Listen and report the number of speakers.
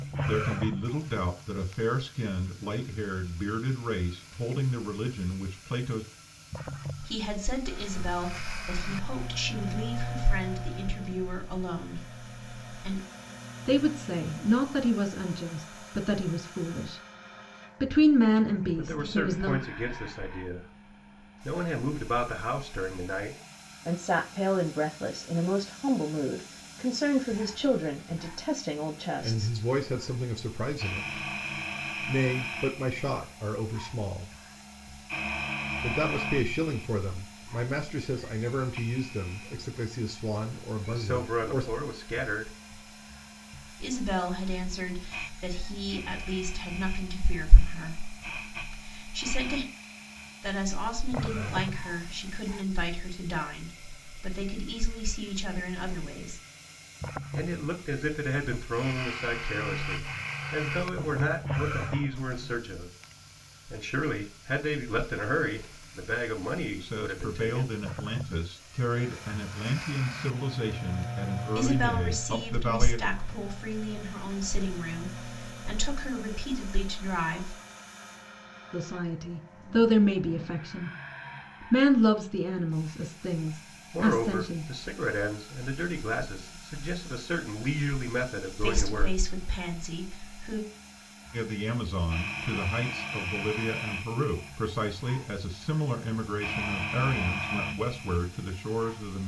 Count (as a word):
six